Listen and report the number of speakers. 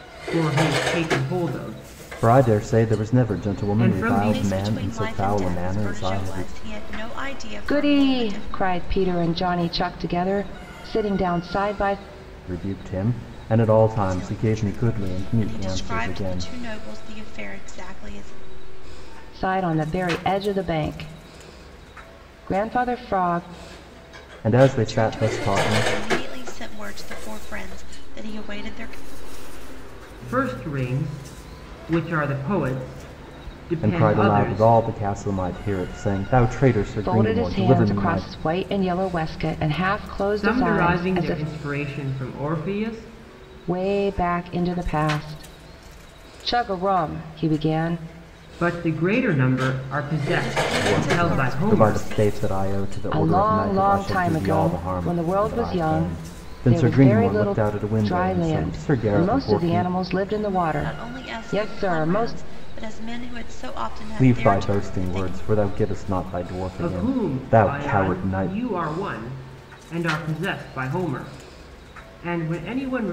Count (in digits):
4